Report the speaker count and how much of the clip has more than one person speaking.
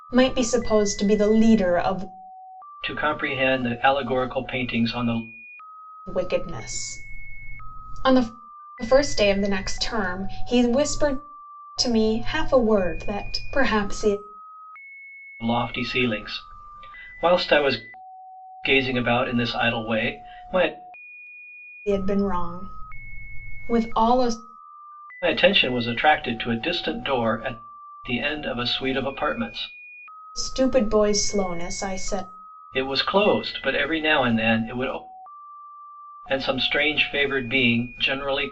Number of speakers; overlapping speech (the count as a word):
two, no overlap